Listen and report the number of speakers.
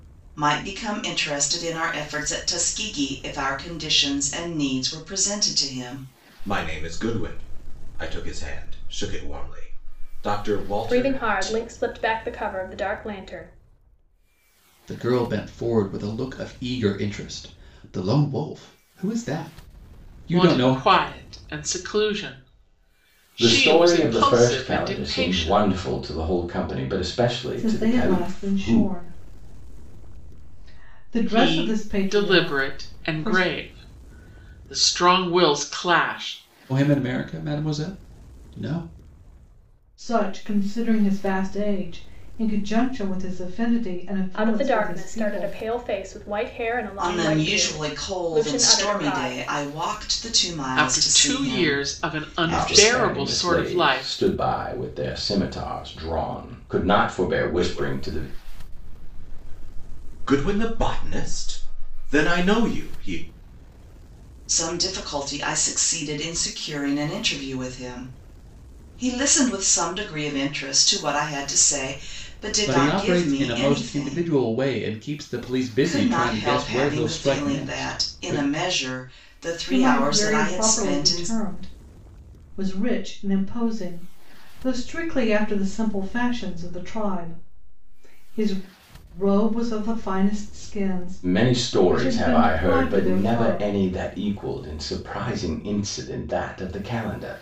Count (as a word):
seven